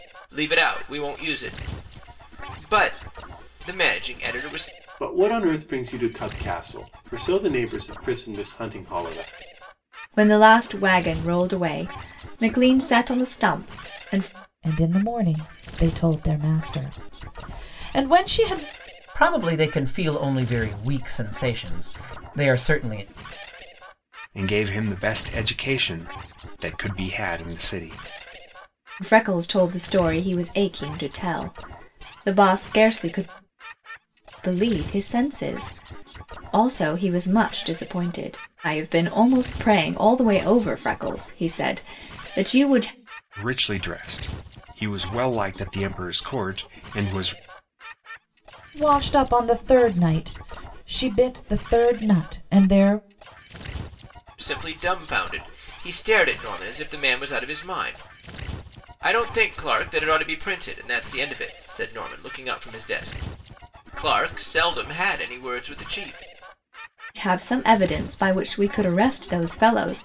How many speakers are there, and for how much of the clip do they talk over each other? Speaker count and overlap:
6, no overlap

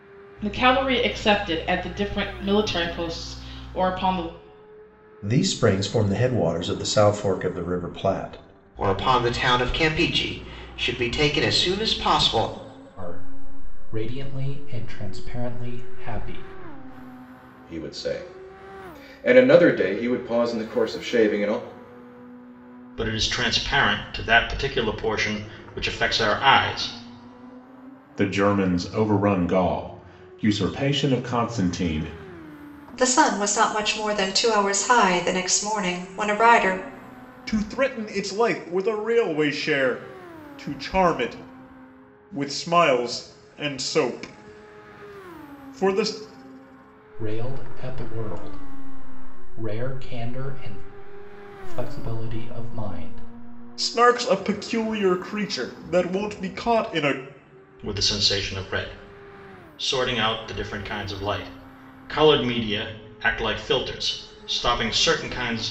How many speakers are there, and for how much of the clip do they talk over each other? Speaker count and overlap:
9, no overlap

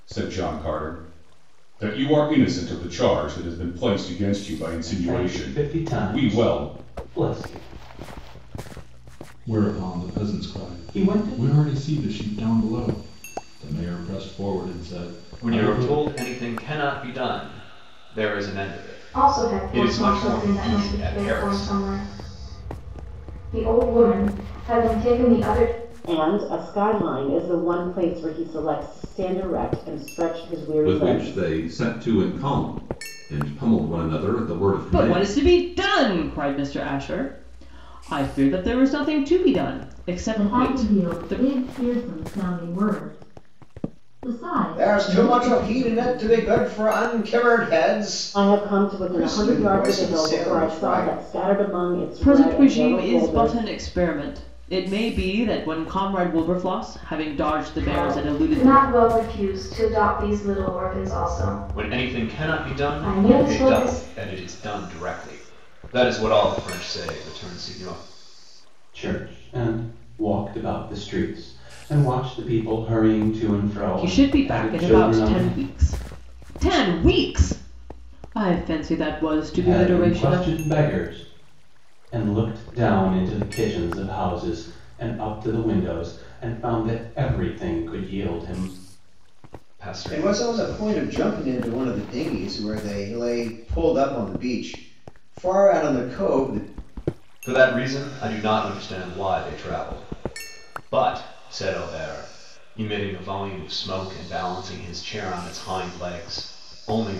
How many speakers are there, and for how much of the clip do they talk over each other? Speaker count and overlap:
10, about 21%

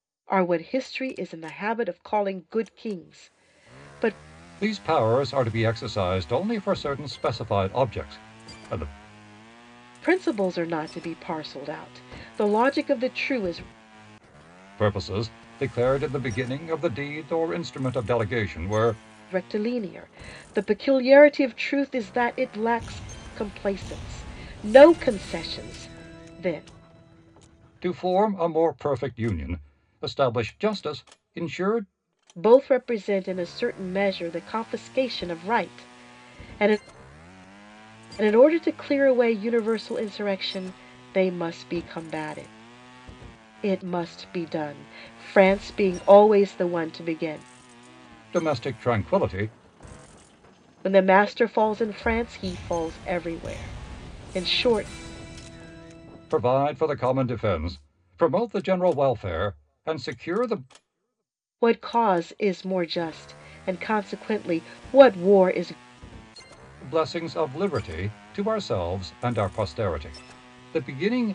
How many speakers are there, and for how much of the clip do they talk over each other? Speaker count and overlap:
2, no overlap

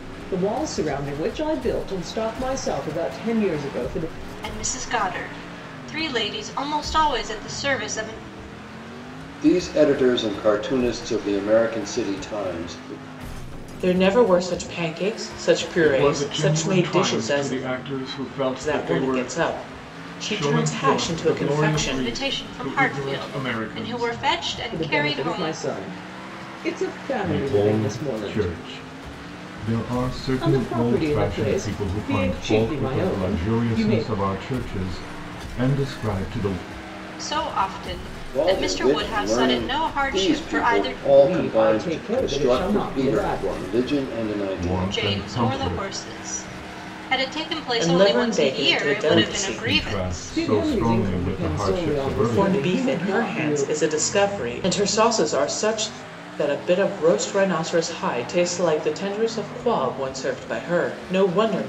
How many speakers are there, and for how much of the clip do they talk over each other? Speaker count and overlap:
5, about 40%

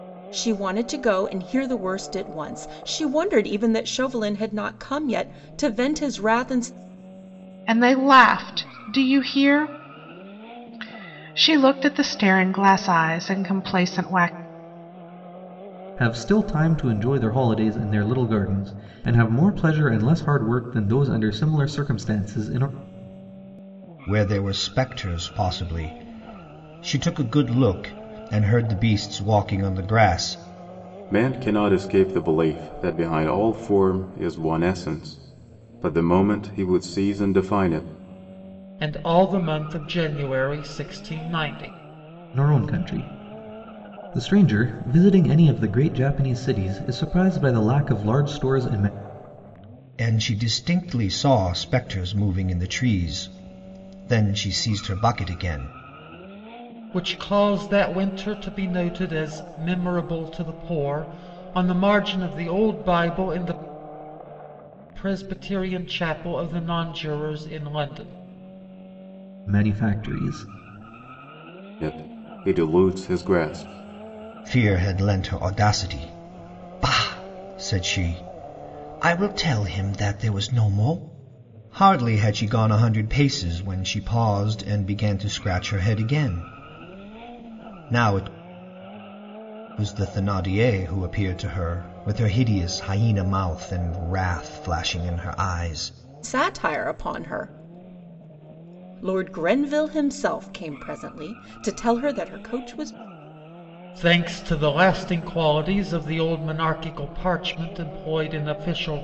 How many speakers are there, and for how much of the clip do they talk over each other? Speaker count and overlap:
6, no overlap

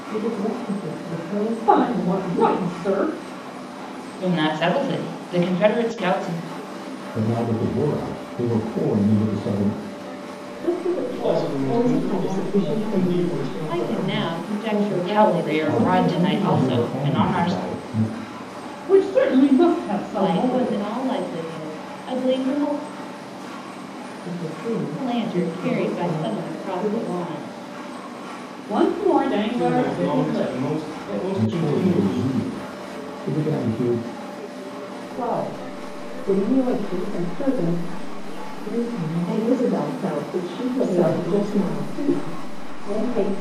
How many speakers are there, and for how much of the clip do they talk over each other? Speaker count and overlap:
8, about 36%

